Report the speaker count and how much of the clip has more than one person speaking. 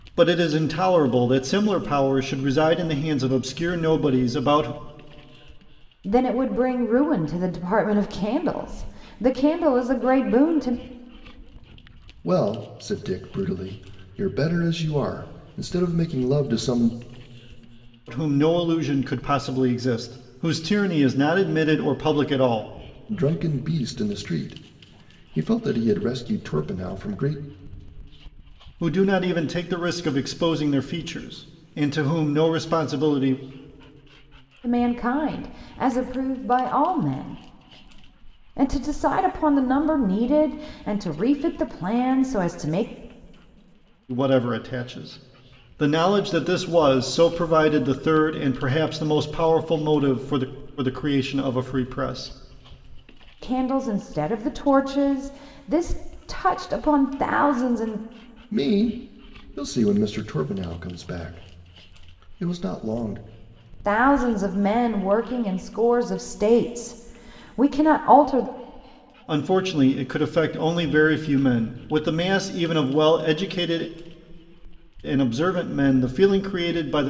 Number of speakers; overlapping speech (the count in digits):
3, no overlap